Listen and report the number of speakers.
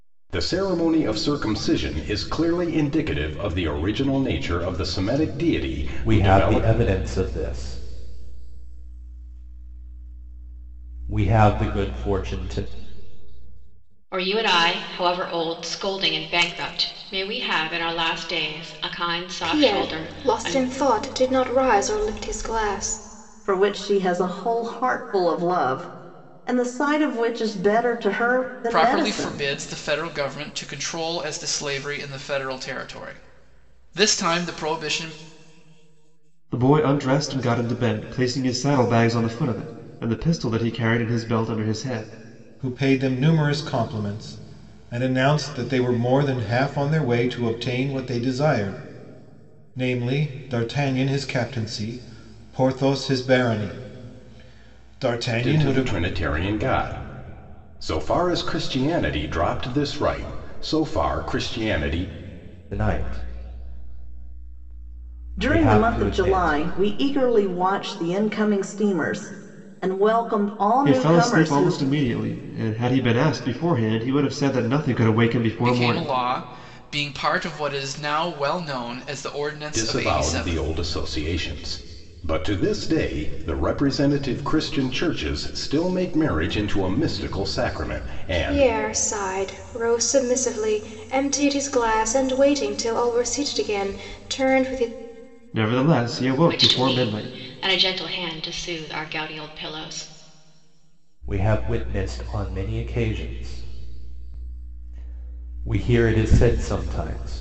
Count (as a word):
eight